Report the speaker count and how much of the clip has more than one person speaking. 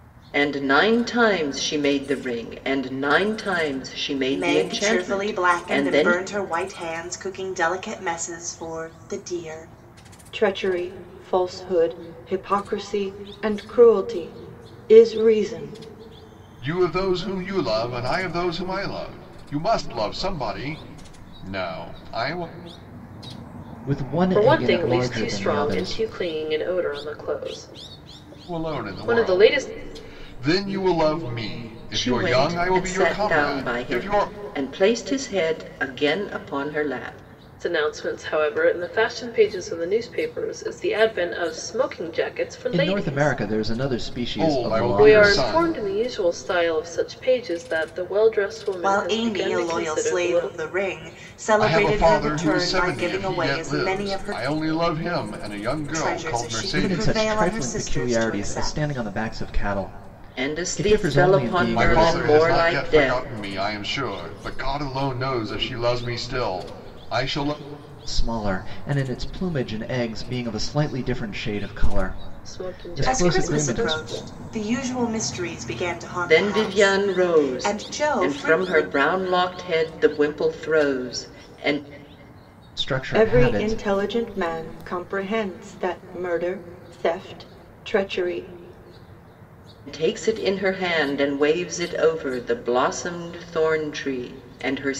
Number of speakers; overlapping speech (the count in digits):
6, about 27%